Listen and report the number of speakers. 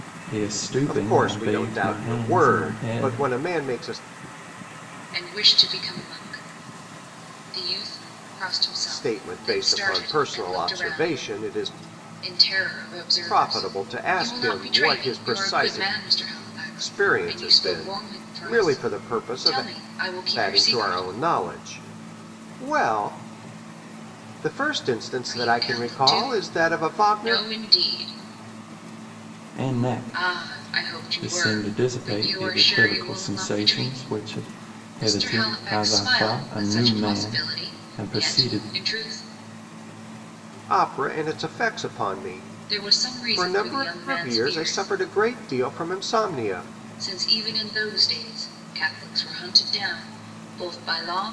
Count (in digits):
3